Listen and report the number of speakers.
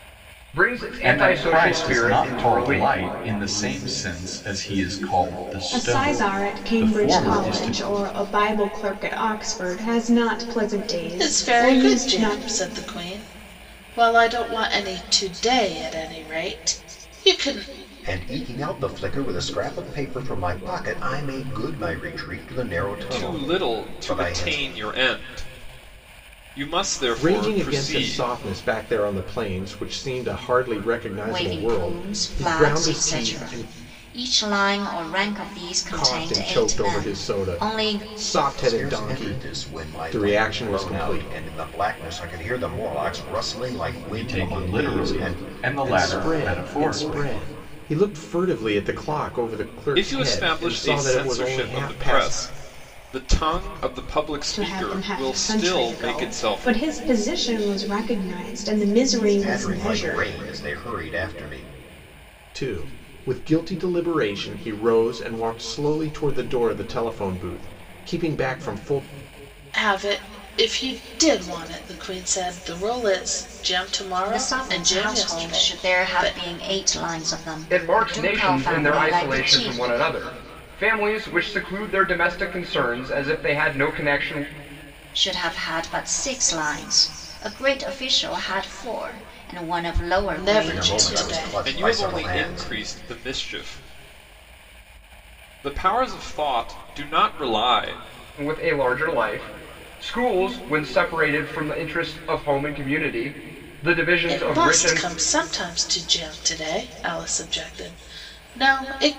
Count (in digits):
8